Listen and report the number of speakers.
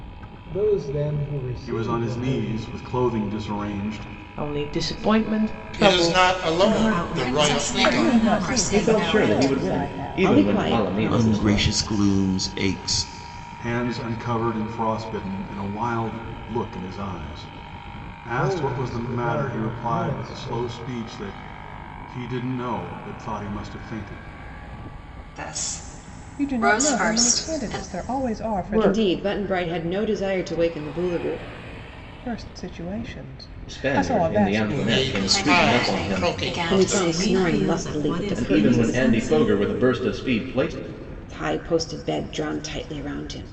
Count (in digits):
10